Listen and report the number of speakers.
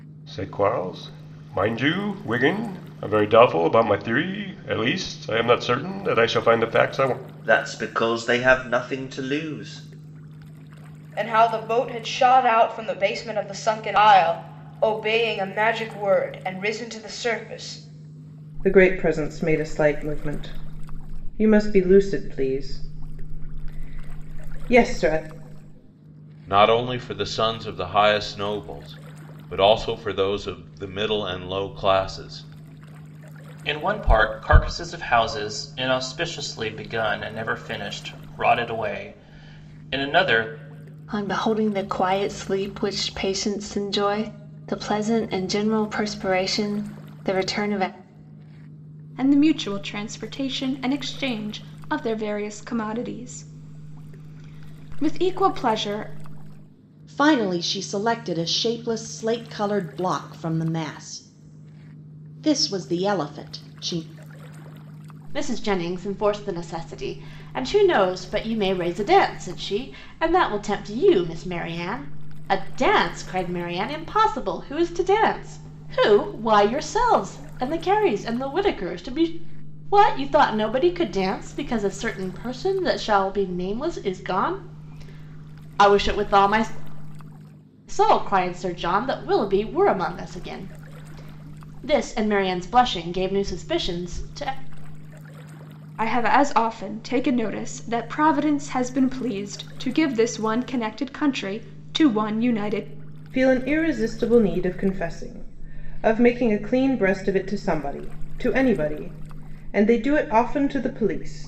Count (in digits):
10